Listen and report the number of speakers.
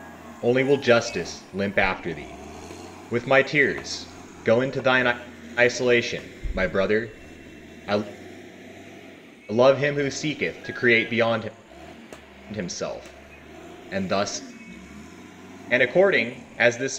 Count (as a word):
one